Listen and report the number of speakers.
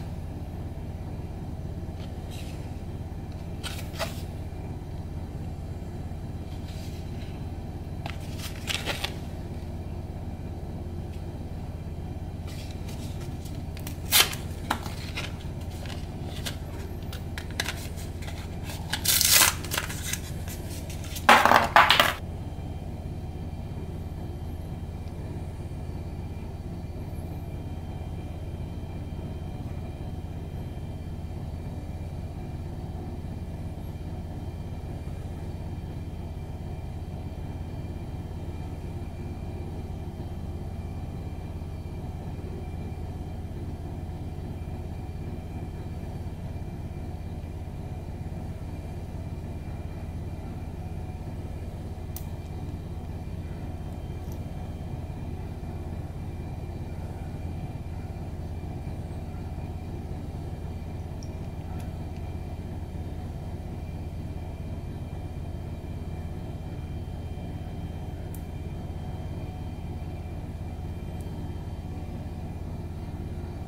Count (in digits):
0